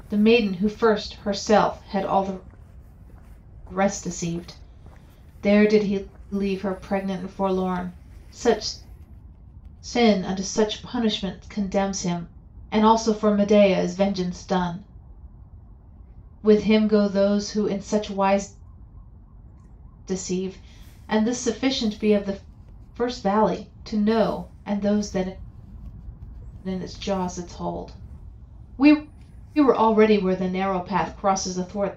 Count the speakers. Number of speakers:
1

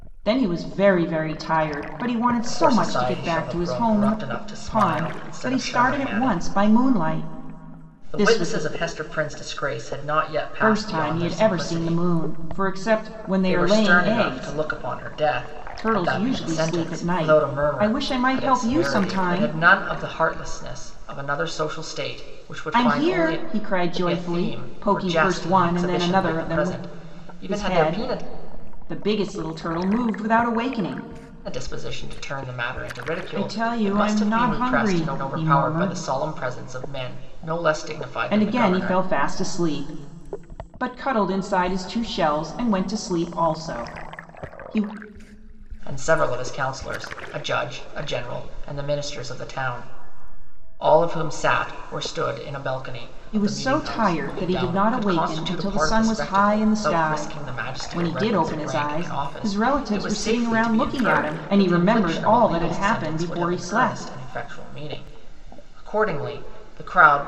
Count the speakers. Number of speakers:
2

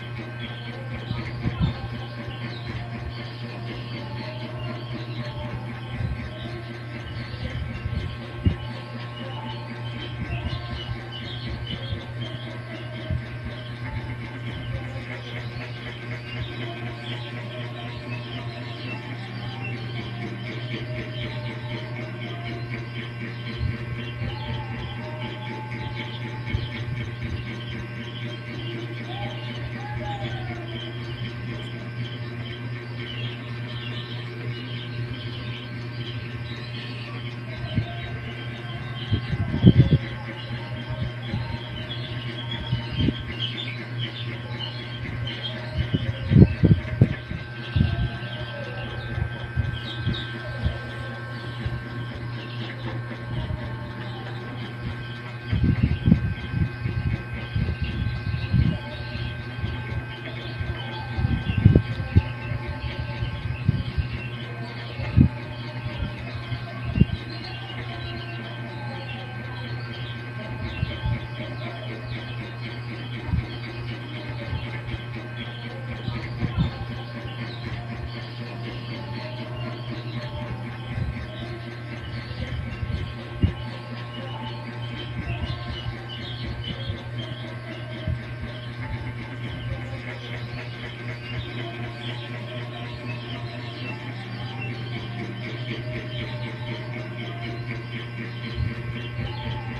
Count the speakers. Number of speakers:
0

